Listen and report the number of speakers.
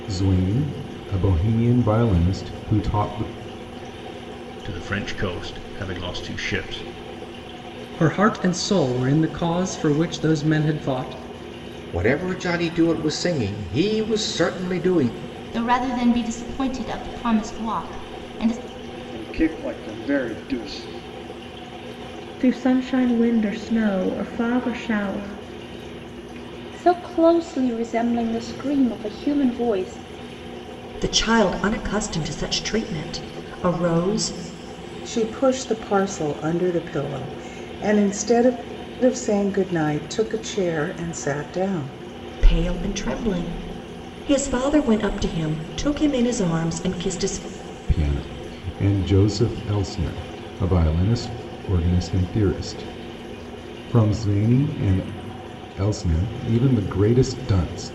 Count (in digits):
10